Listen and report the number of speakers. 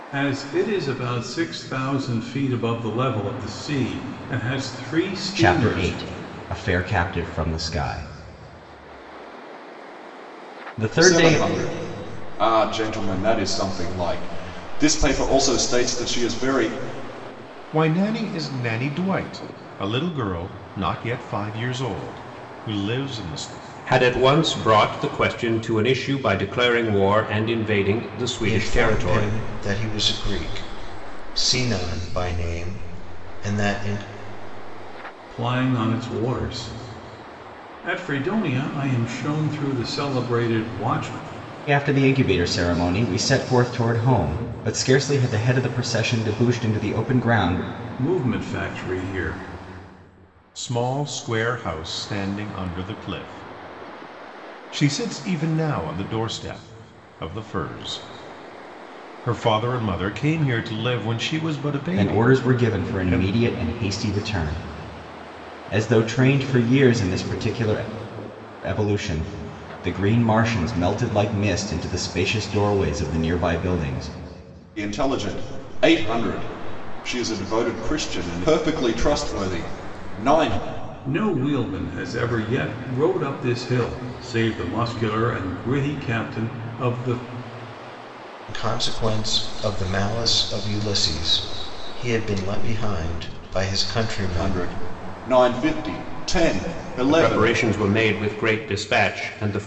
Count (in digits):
6